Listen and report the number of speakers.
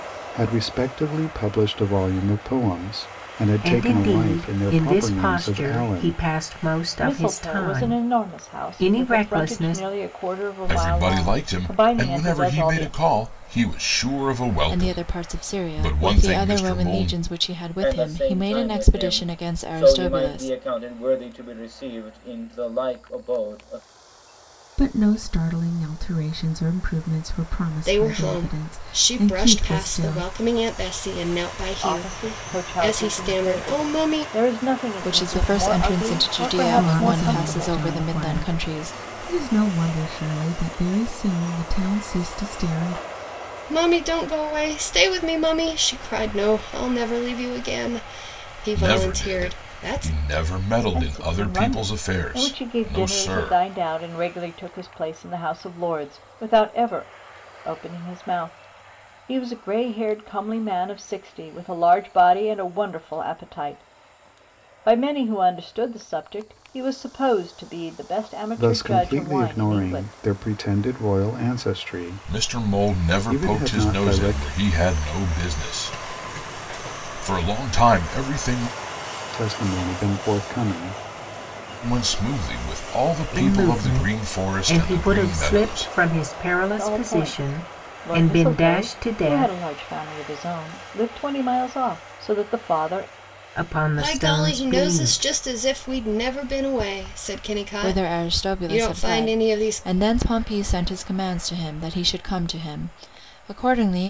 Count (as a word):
eight